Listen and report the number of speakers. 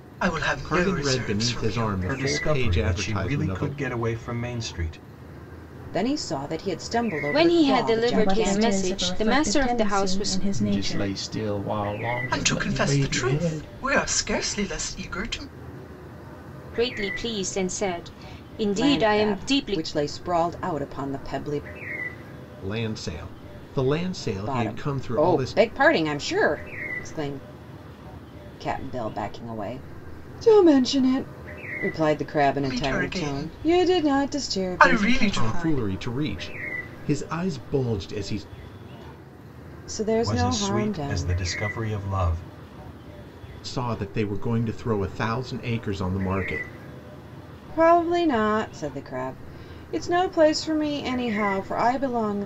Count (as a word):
seven